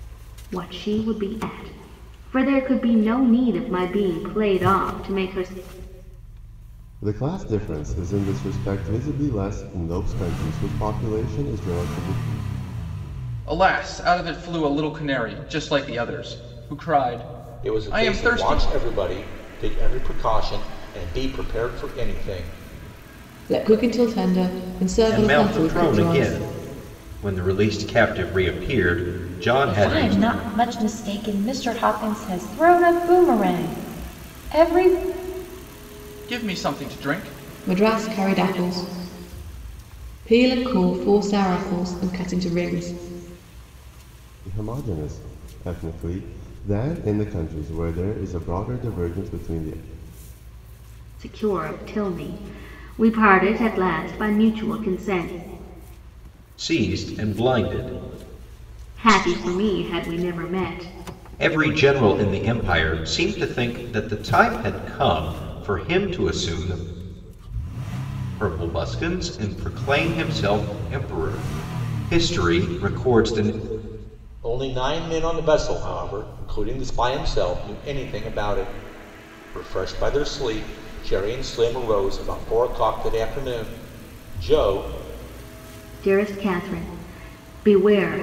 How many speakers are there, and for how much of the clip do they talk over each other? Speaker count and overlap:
seven, about 3%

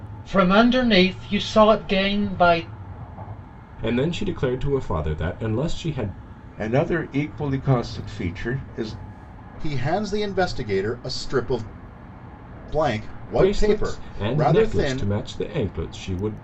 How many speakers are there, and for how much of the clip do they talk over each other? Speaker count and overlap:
four, about 11%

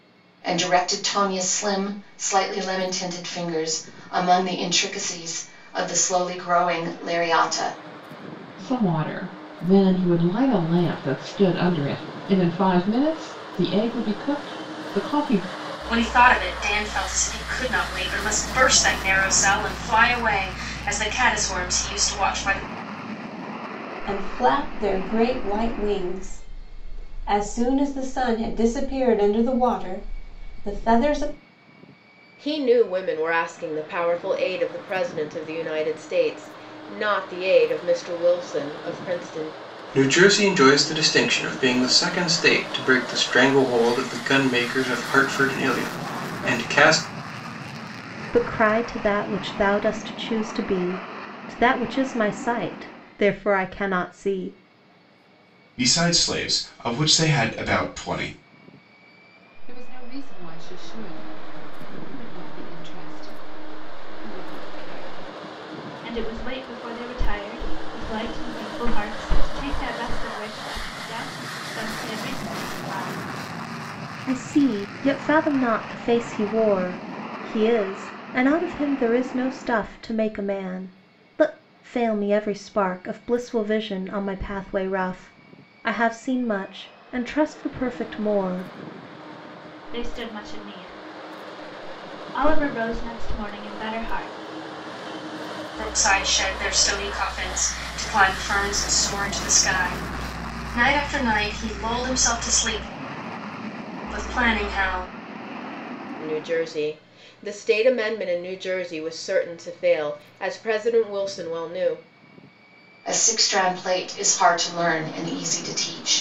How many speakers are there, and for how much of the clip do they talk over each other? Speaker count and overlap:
ten, no overlap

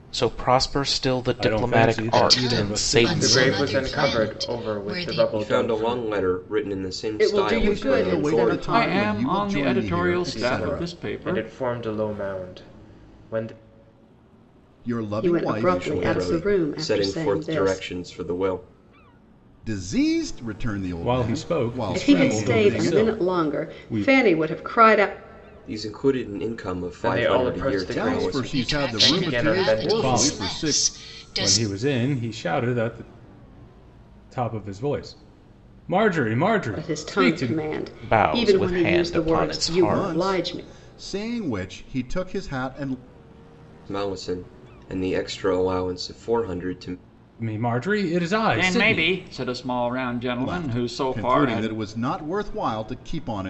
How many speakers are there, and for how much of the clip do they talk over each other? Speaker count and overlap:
eight, about 47%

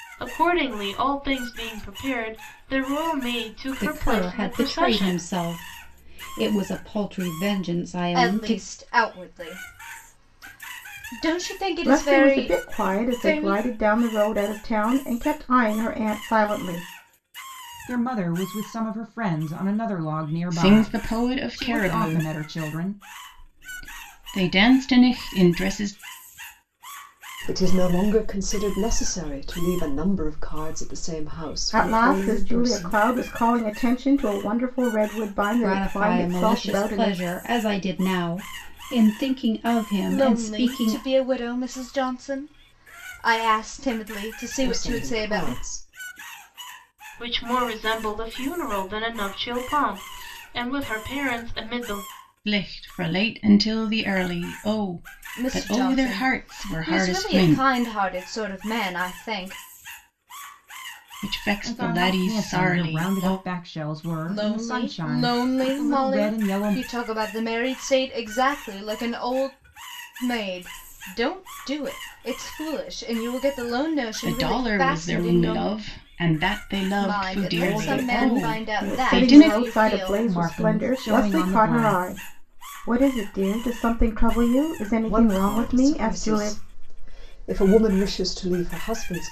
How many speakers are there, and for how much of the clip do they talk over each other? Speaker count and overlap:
seven, about 29%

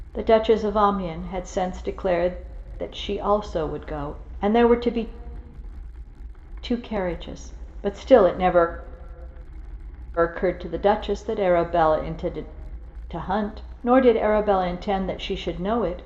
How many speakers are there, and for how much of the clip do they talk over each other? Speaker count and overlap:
one, no overlap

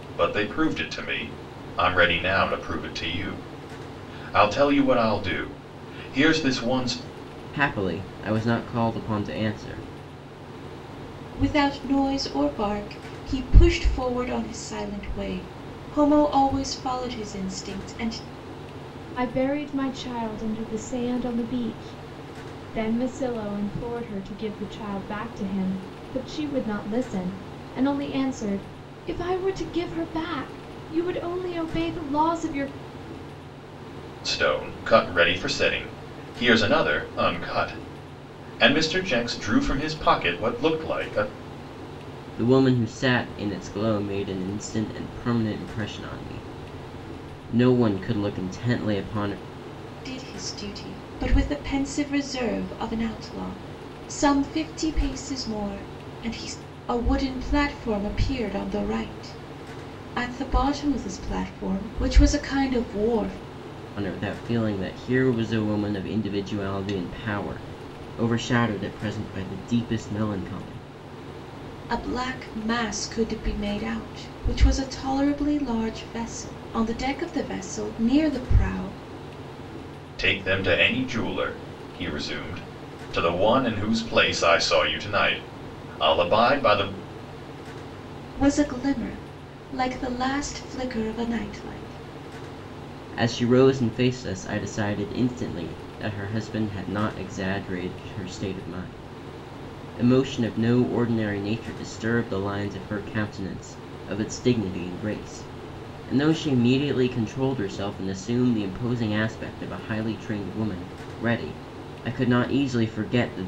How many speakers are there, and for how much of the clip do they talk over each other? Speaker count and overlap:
four, no overlap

